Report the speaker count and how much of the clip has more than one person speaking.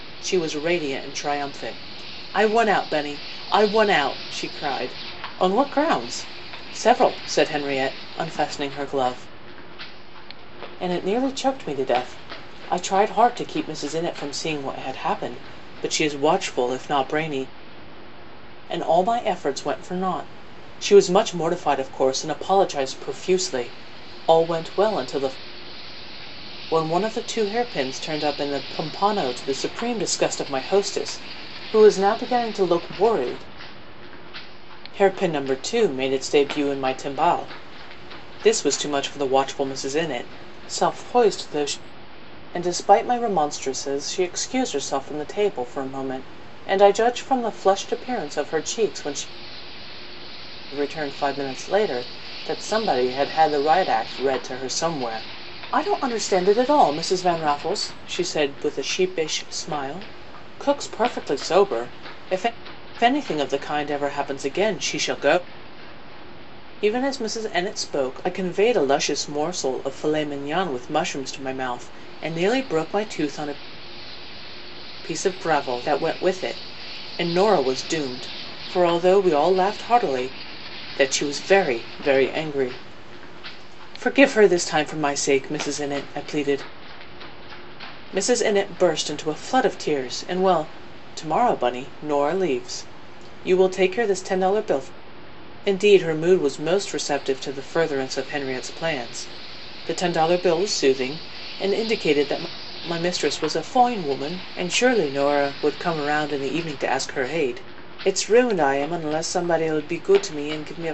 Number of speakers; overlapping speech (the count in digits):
1, no overlap